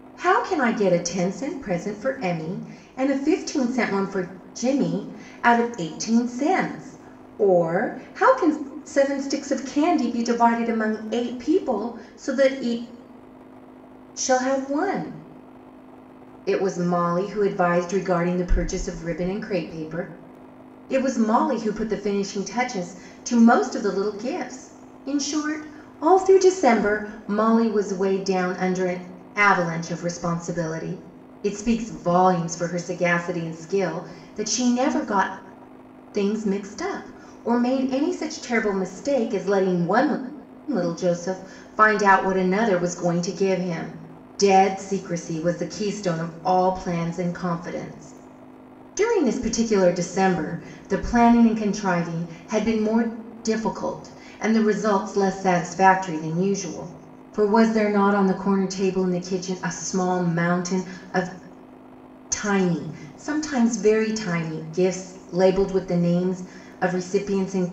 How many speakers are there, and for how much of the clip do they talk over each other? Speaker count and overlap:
one, no overlap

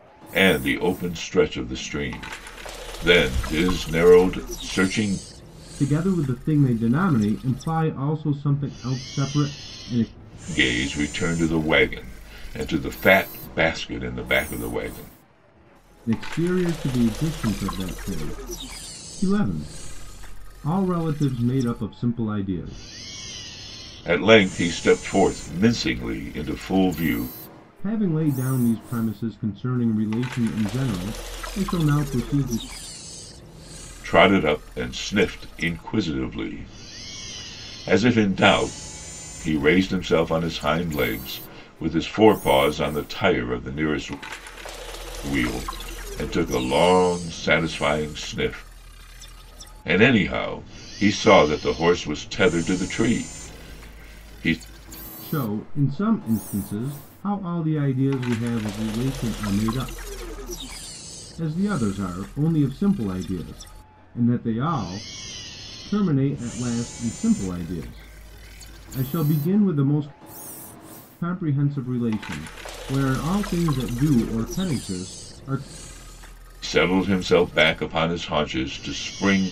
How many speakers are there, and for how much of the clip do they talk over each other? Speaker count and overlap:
two, no overlap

